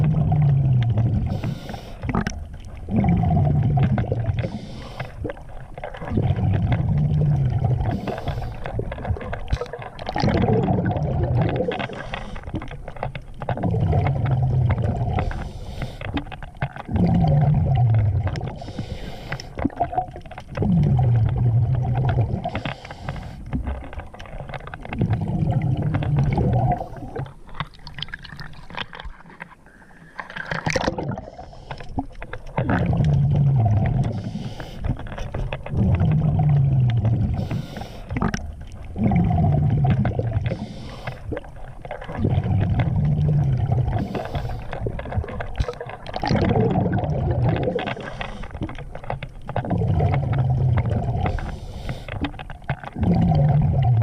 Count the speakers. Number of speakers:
0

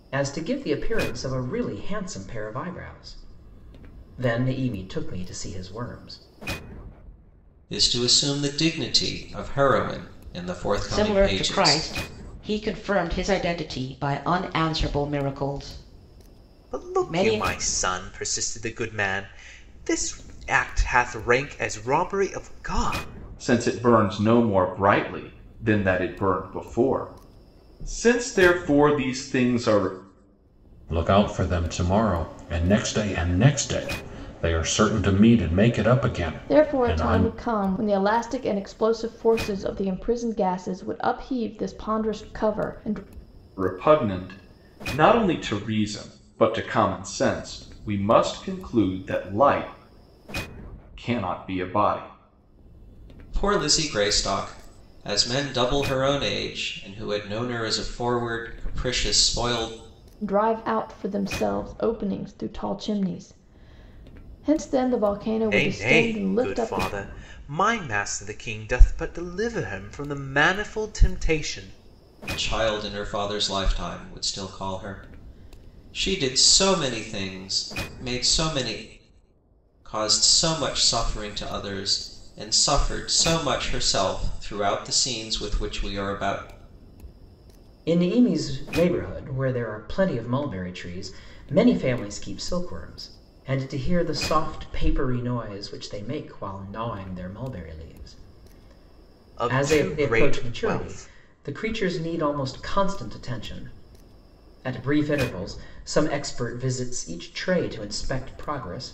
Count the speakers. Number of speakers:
7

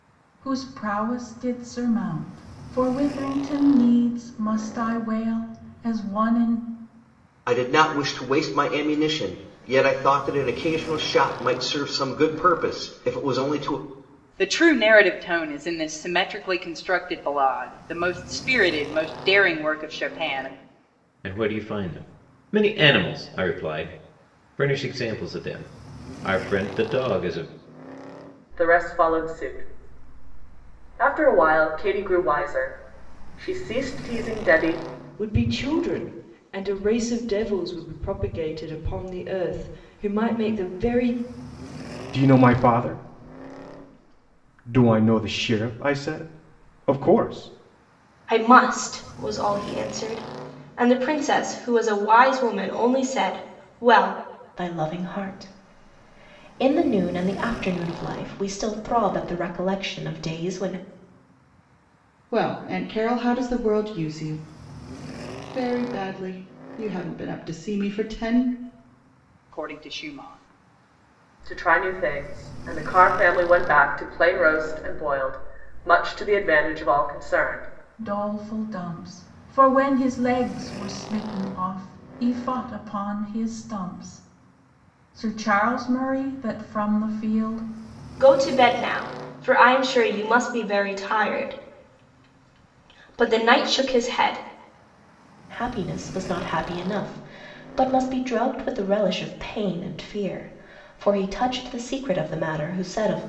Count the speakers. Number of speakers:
10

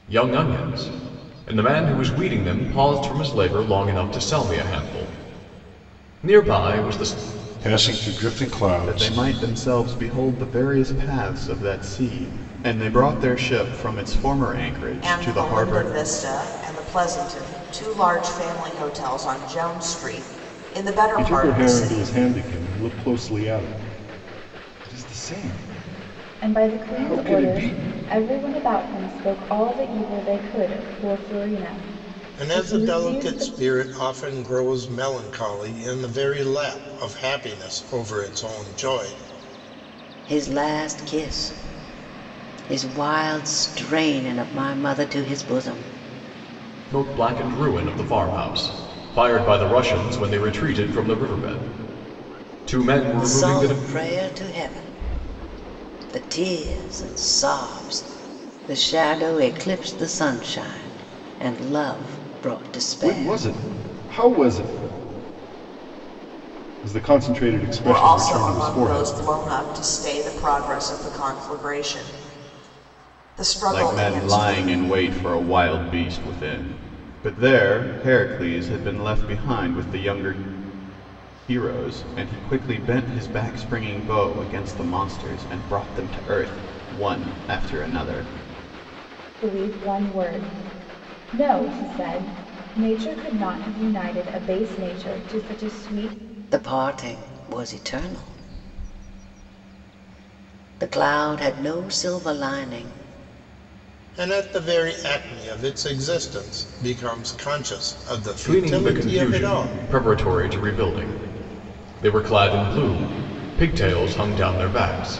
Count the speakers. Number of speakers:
8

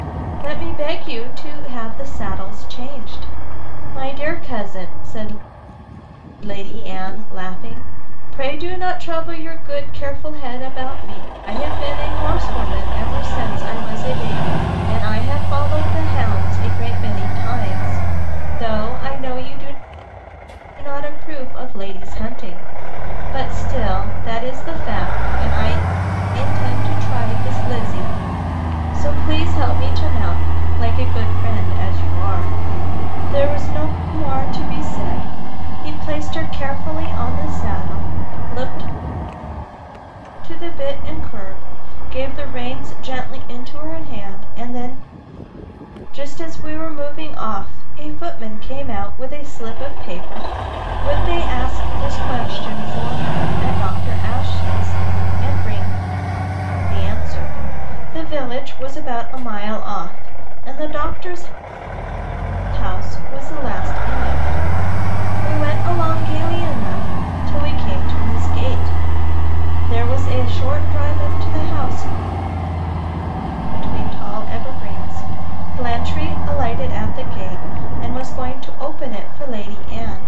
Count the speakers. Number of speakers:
1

